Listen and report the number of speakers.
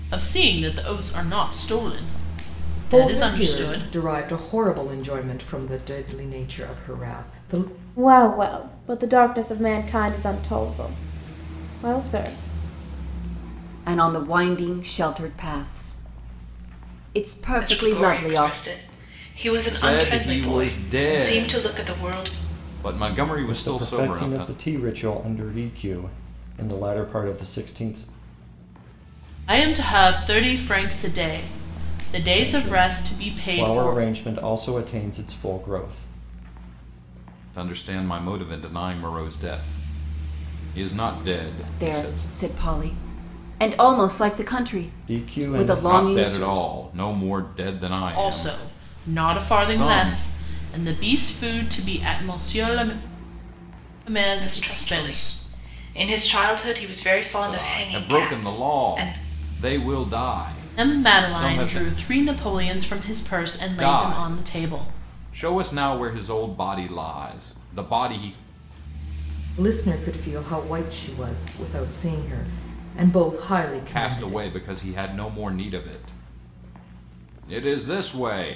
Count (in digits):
7